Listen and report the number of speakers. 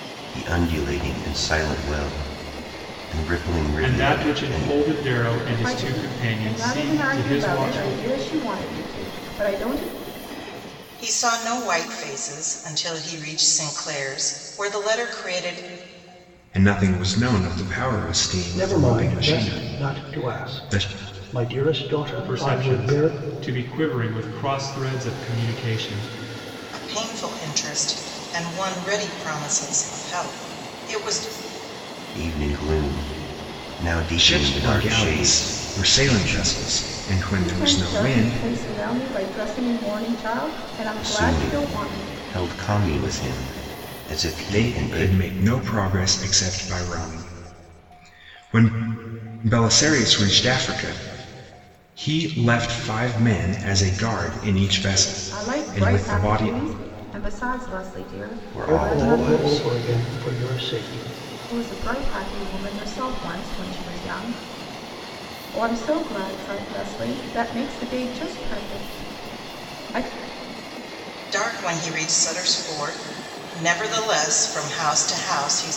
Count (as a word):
six